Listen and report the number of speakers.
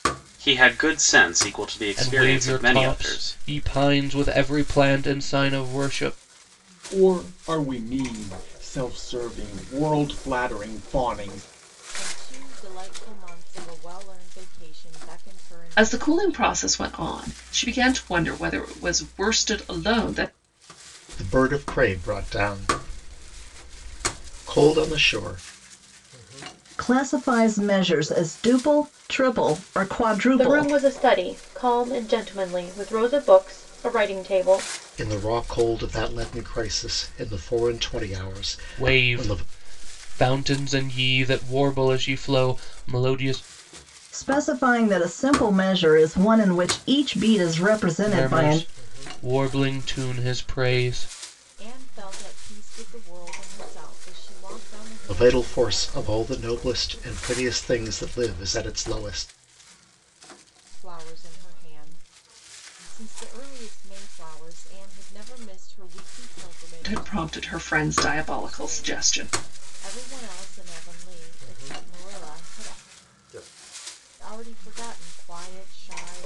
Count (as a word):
eight